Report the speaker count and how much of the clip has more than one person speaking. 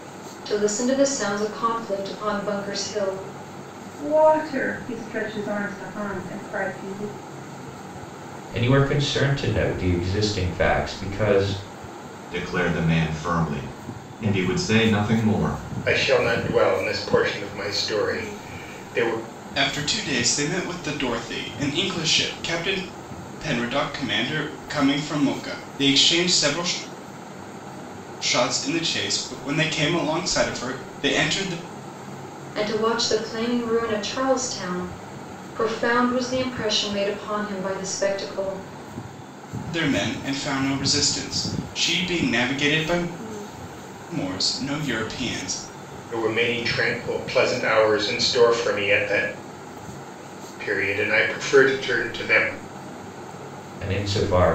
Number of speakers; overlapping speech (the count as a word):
six, no overlap